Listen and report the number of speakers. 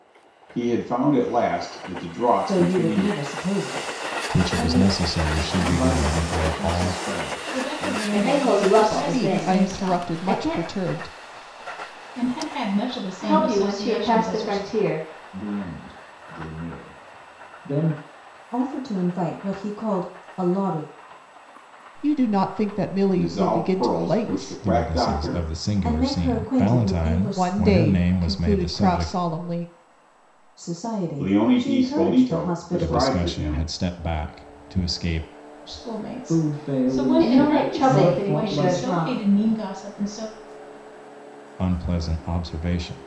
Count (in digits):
7